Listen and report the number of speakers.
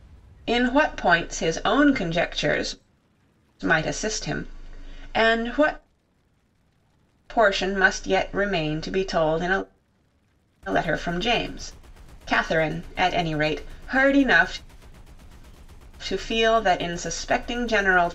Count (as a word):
one